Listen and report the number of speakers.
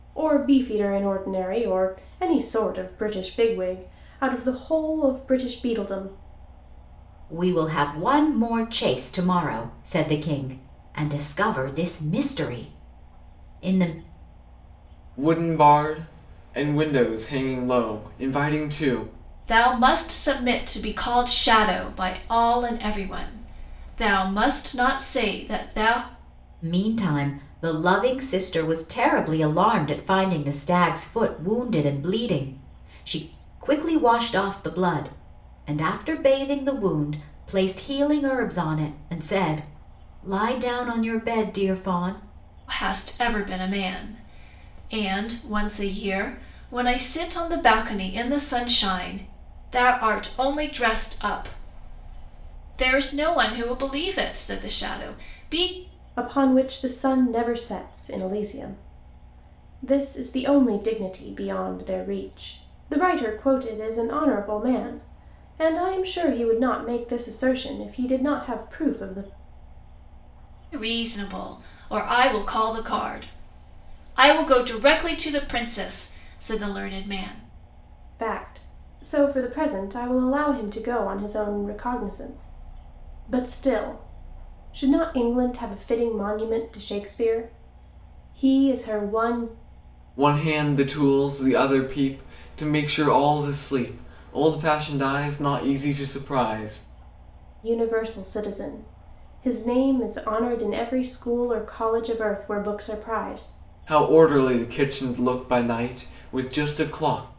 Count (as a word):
four